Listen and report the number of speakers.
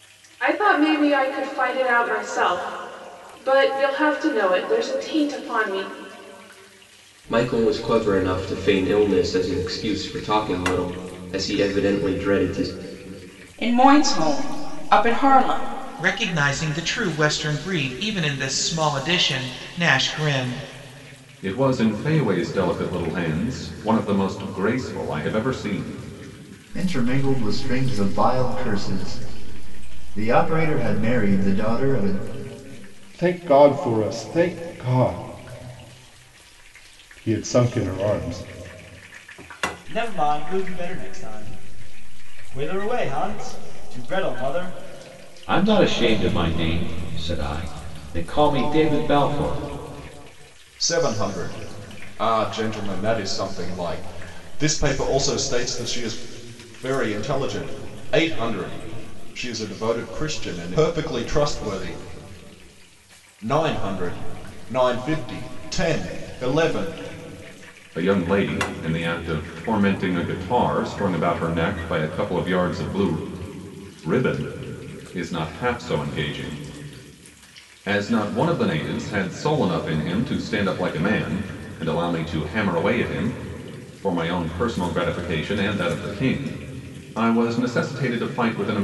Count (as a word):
ten